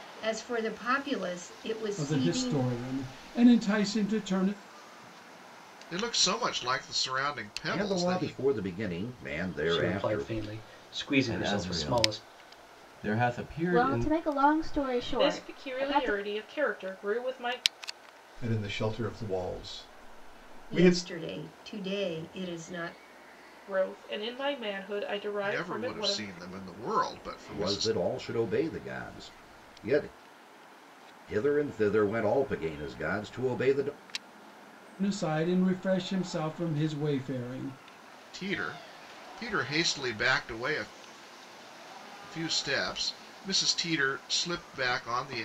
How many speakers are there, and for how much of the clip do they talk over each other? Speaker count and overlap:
nine, about 14%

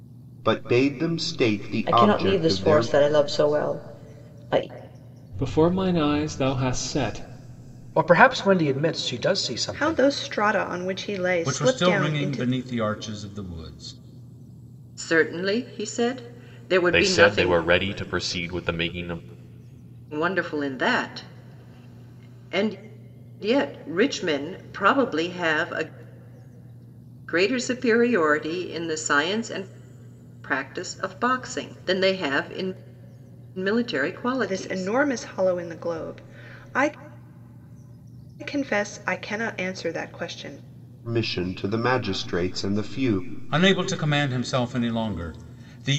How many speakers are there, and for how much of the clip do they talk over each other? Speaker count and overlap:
eight, about 8%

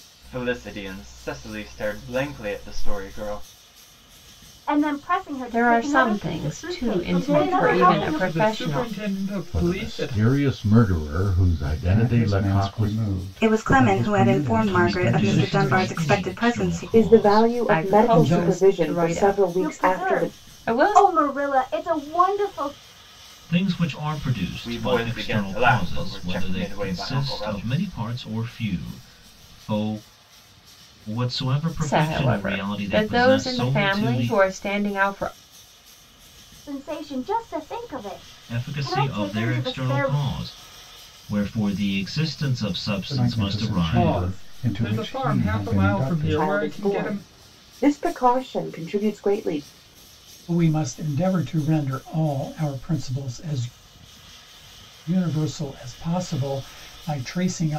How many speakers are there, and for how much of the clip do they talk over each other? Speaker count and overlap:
ten, about 43%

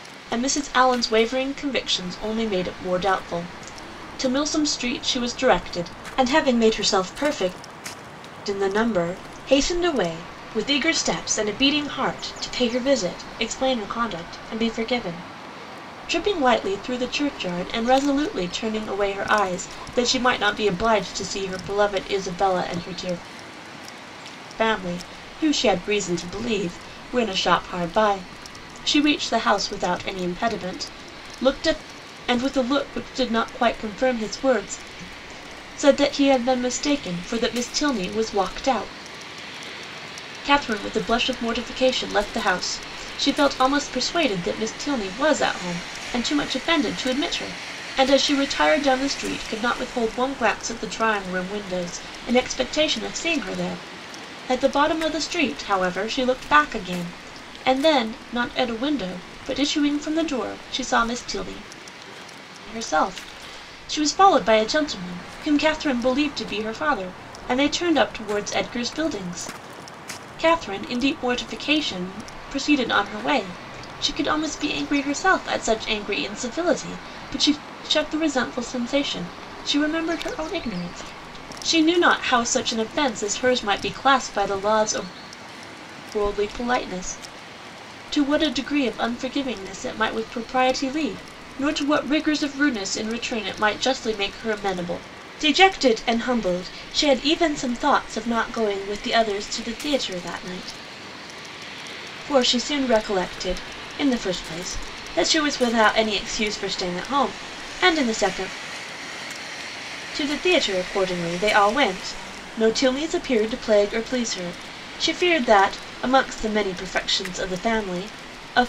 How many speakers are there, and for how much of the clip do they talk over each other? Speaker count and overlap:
one, no overlap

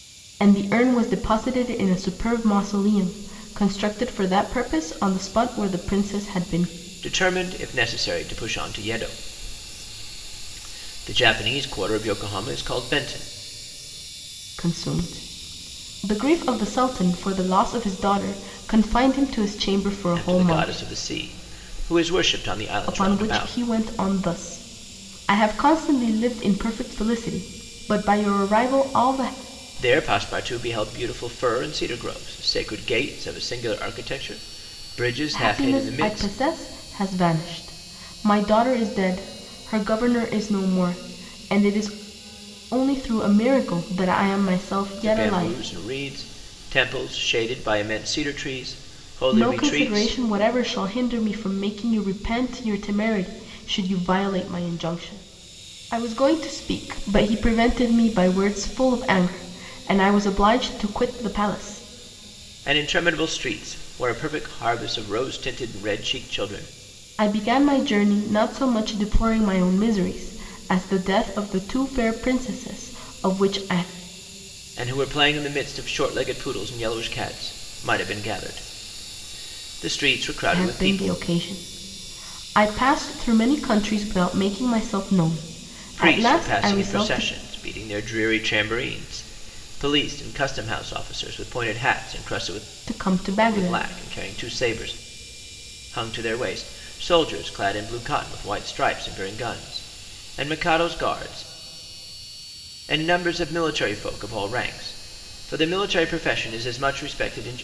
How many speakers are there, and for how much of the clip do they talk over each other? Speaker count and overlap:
two, about 6%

